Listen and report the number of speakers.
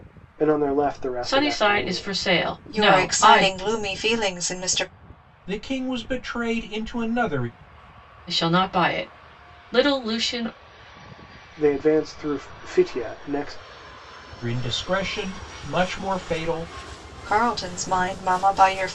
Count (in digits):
4